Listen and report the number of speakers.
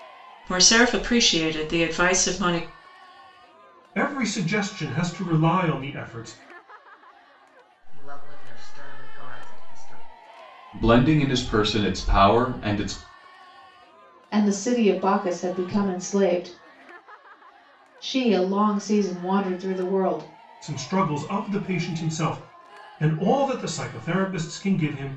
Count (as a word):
five